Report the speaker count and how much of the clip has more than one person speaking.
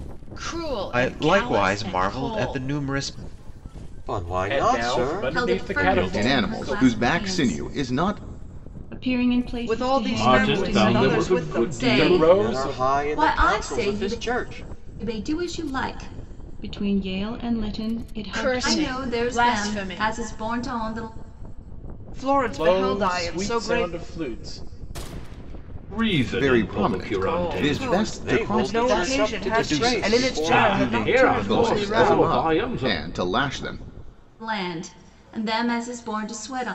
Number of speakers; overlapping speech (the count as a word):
nine, about 53%